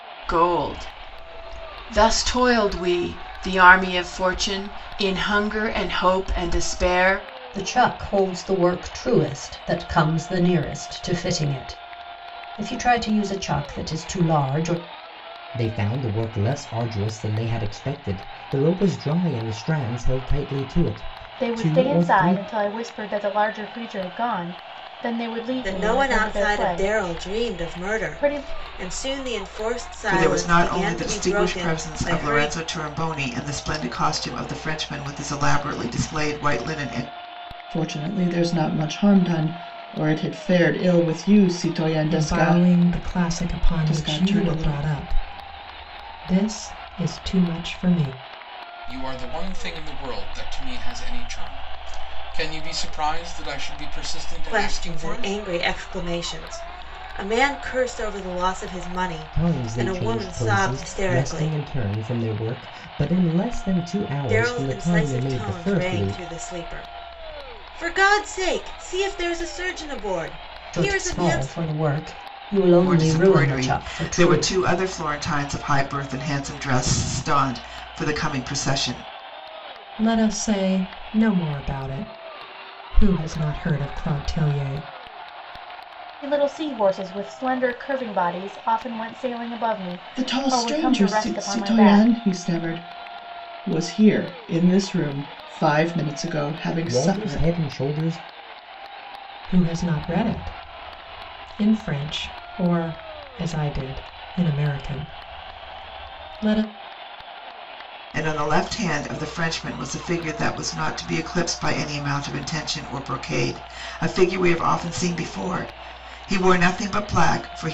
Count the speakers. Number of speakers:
nine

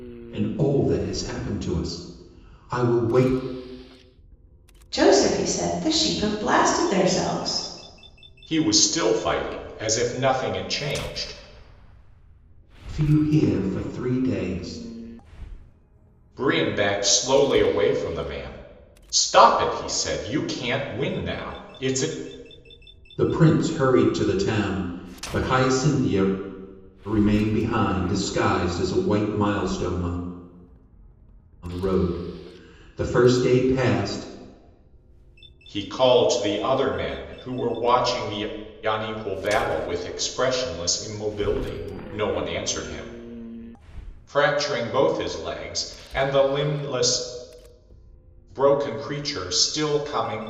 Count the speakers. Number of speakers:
three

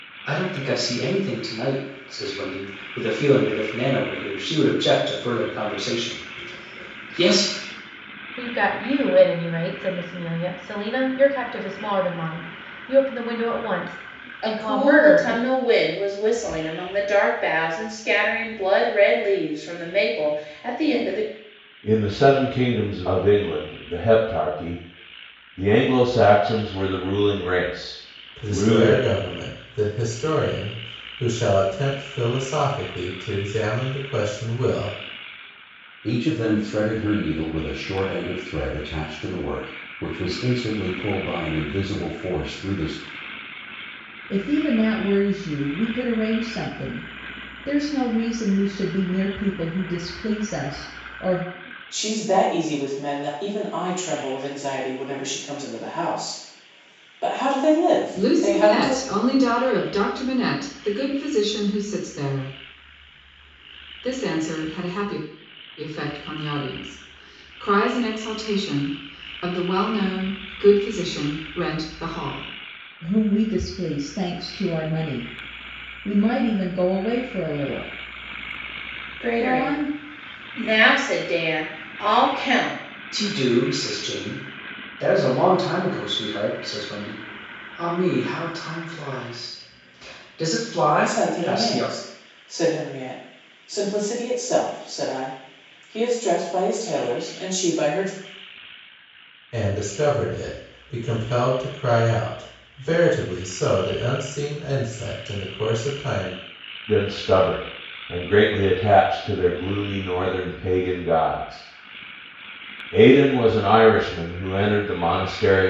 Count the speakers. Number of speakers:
nine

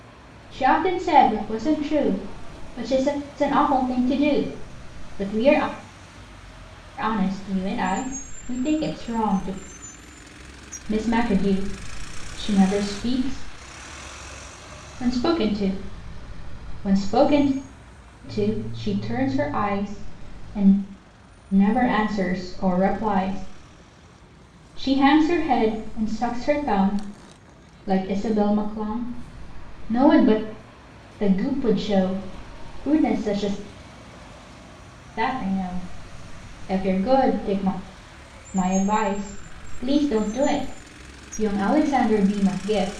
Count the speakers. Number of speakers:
one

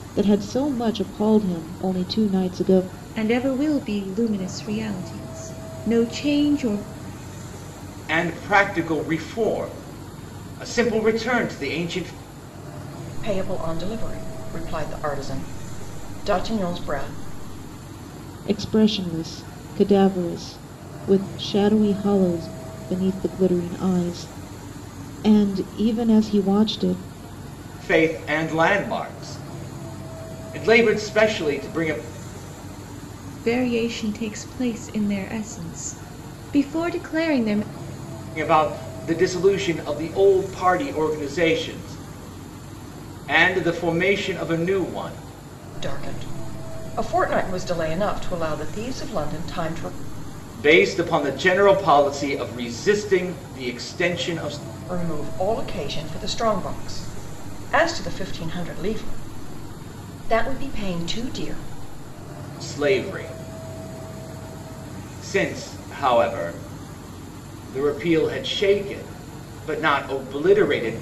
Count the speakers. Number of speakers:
four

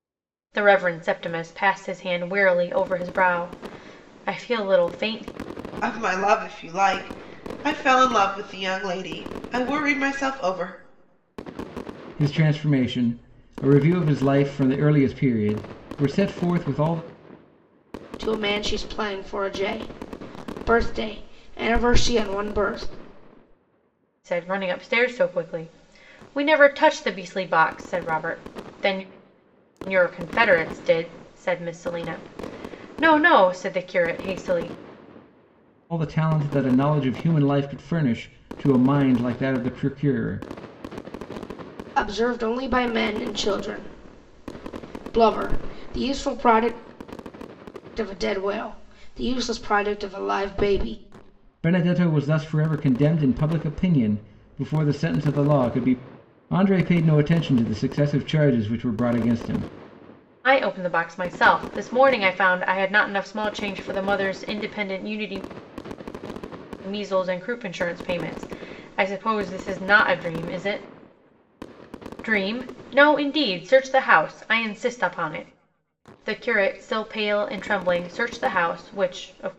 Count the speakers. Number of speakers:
four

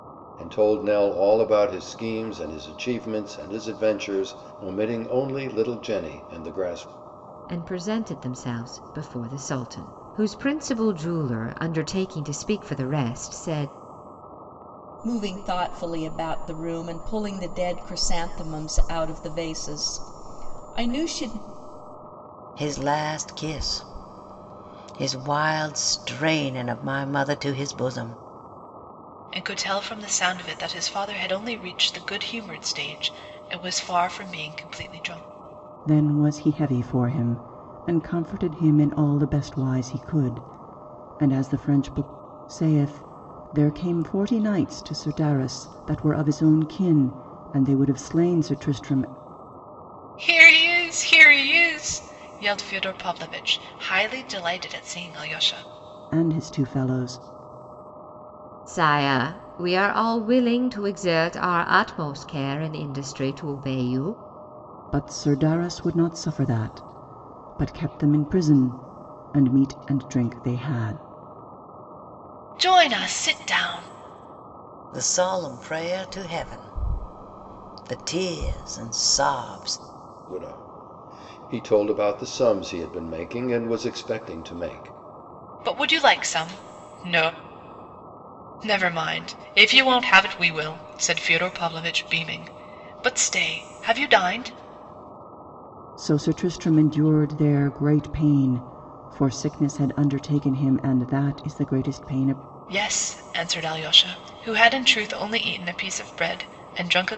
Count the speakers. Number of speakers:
six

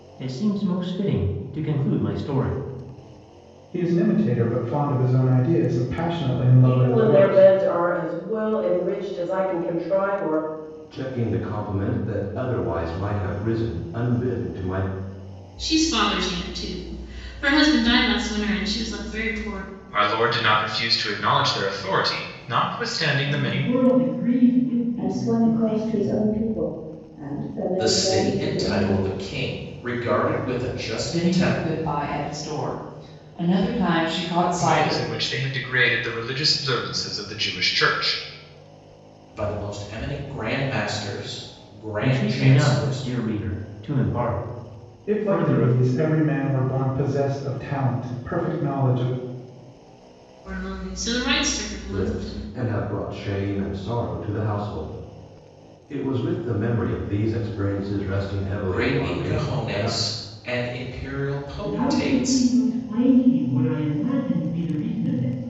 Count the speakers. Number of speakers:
ten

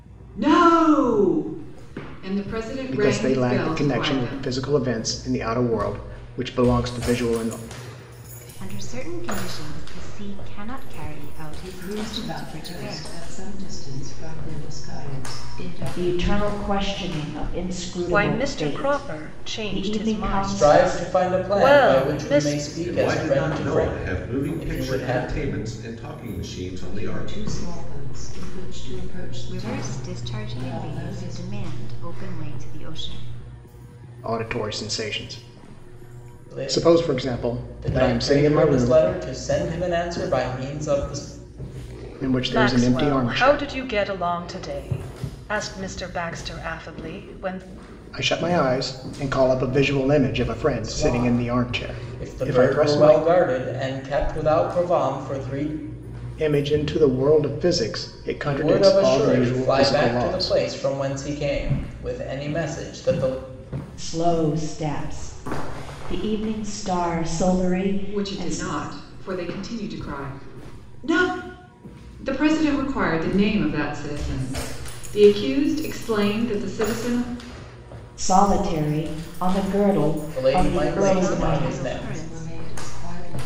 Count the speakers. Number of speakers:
eight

